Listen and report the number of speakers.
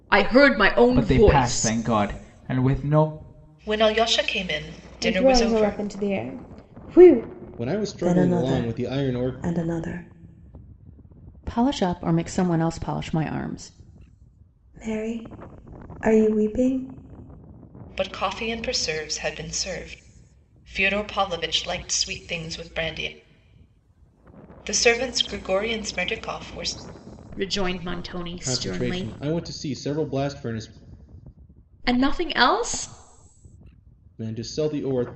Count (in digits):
7